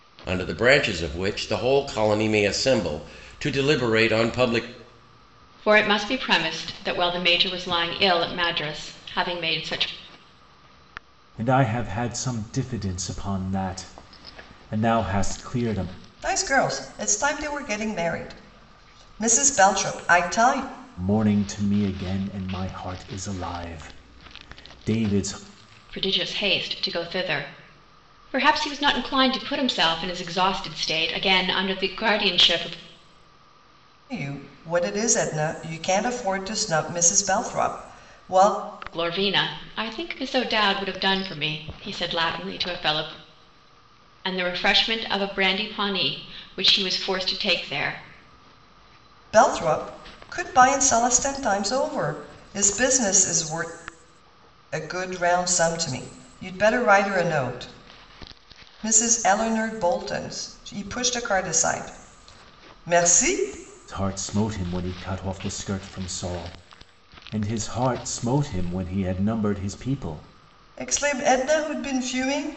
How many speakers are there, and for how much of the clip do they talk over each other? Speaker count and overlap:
4, no overlap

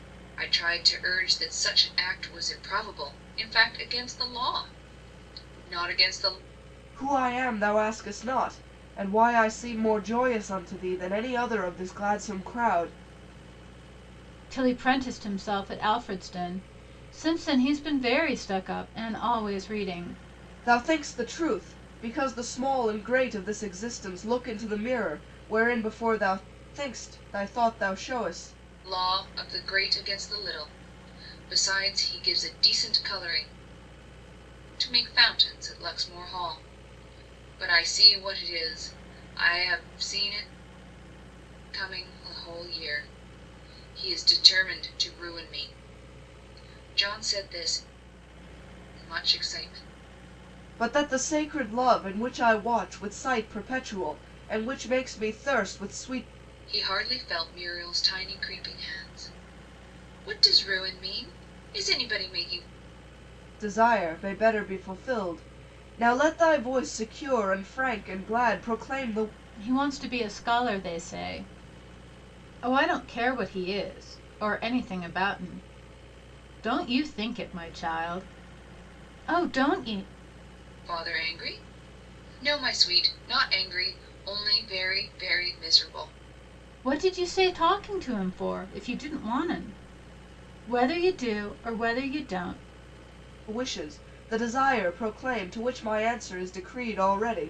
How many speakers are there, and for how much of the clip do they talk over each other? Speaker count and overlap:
3, no overlap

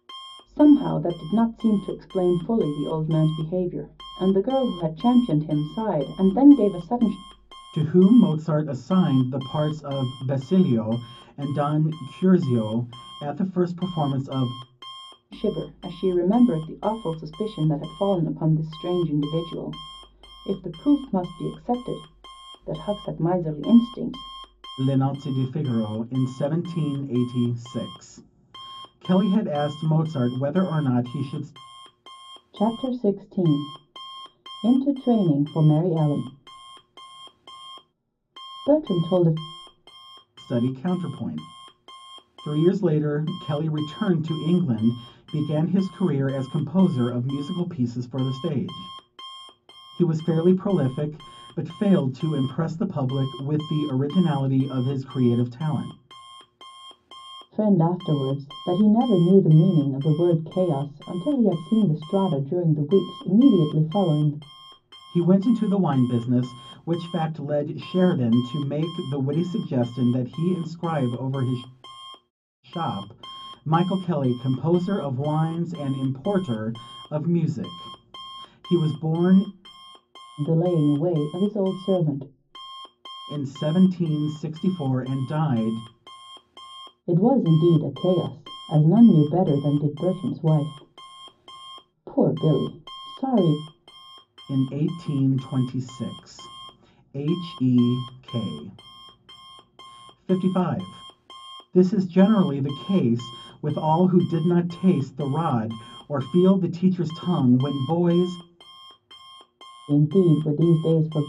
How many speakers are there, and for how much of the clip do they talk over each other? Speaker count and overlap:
2, no overlap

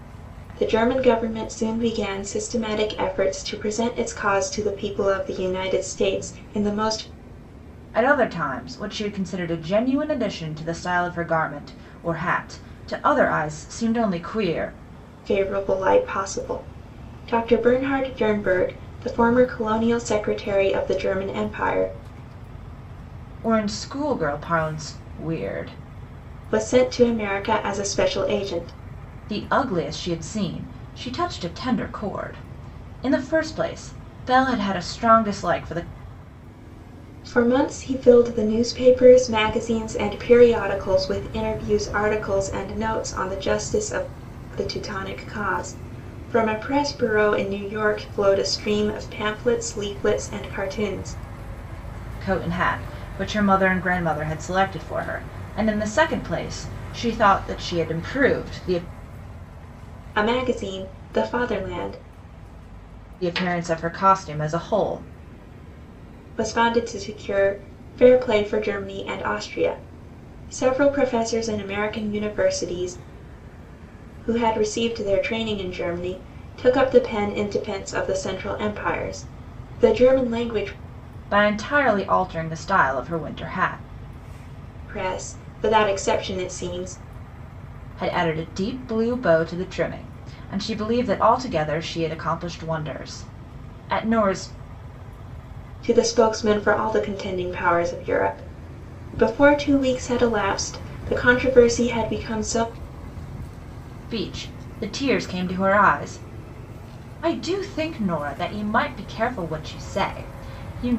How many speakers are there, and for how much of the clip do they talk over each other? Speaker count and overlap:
2, no overlap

